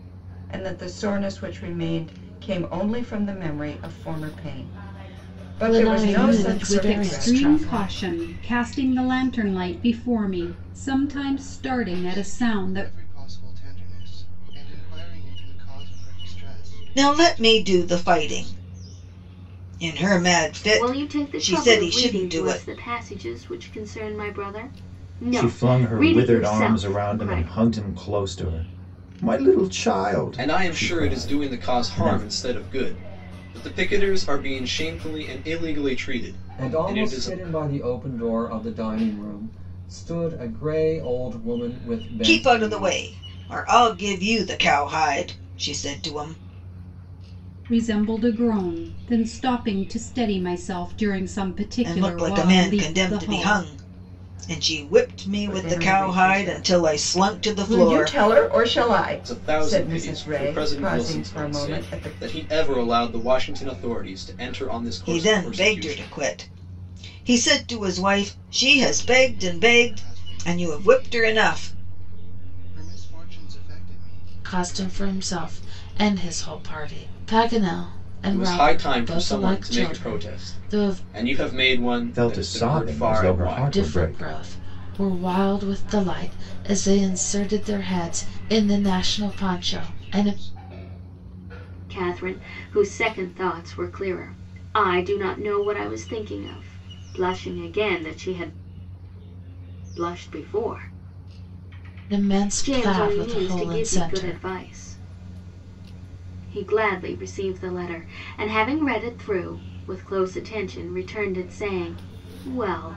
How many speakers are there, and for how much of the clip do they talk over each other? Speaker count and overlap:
9, about 30%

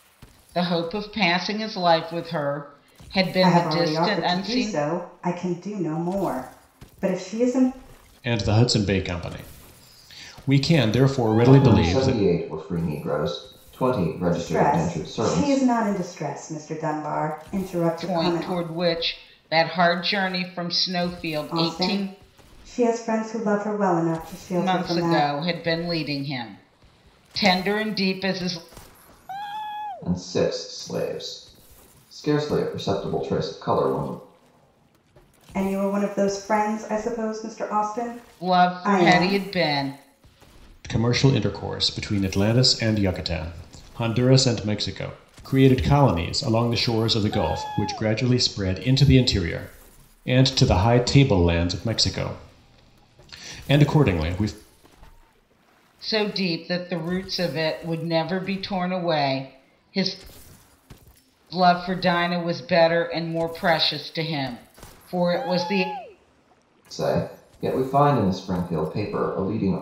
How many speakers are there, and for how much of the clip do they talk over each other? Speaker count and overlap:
4, about 9%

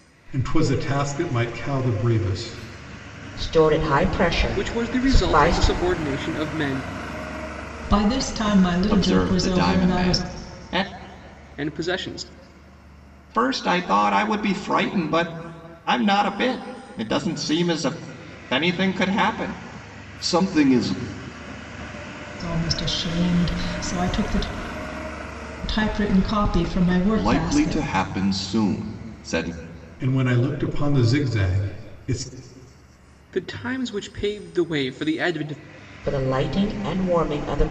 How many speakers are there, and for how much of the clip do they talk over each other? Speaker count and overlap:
5, about 9%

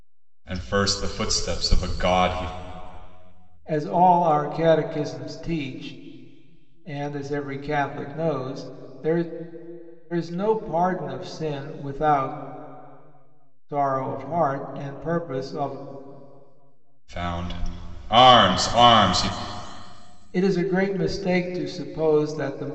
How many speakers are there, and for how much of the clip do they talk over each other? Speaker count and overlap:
2, no overlap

